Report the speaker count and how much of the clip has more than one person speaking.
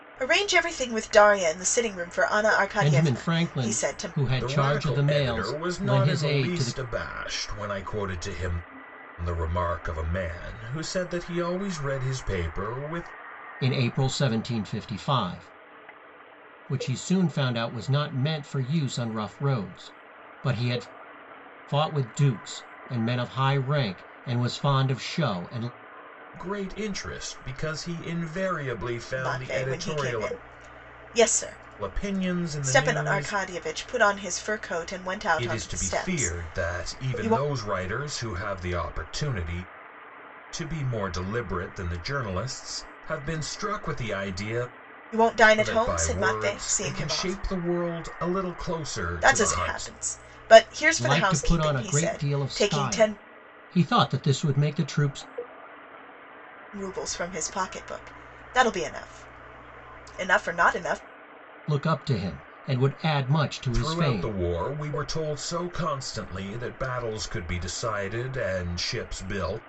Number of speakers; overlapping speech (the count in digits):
3, about 20%